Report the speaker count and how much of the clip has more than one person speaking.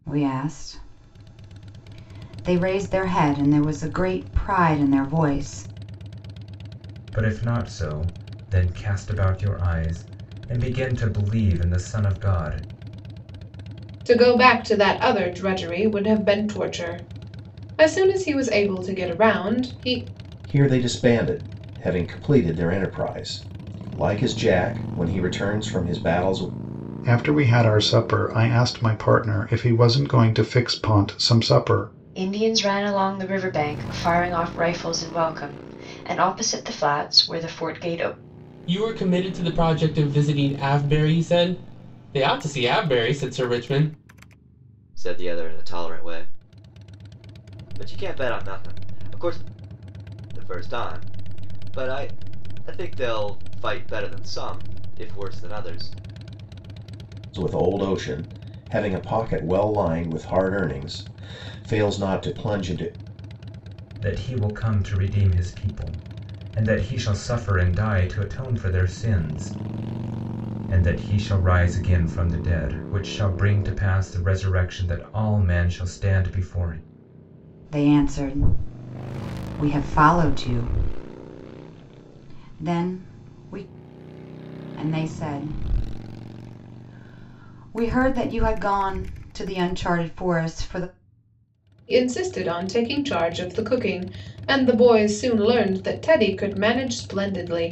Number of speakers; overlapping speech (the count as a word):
eight, no overlap